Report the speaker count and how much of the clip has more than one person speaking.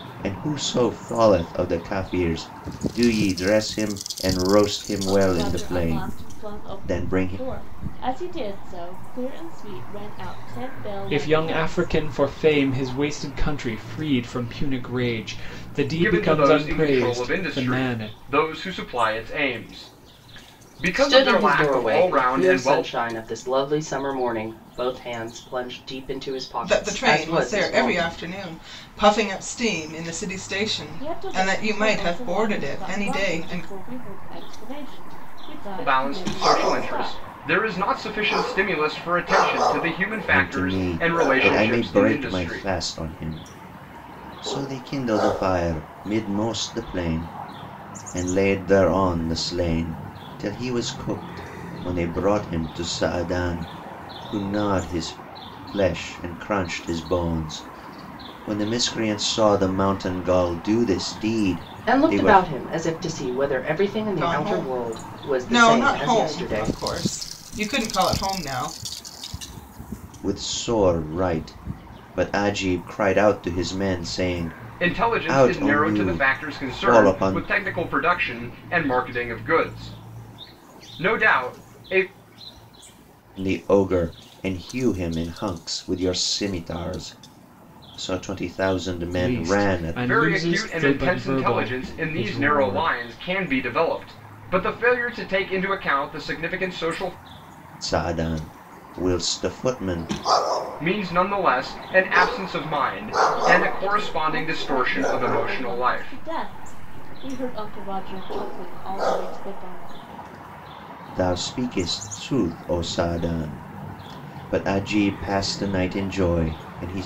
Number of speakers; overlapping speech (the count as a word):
six, about 24%